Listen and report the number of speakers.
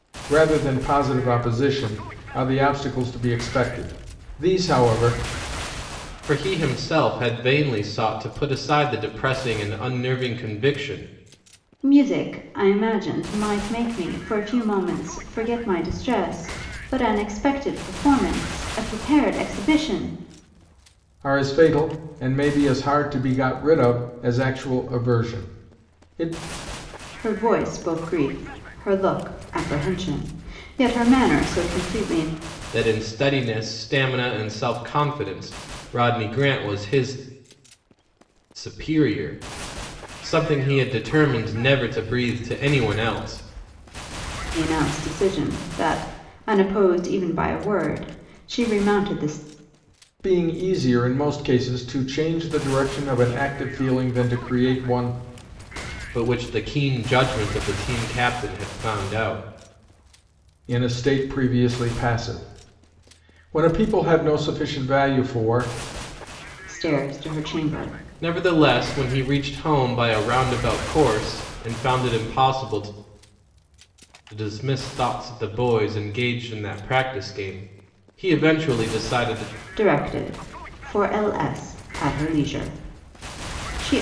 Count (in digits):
3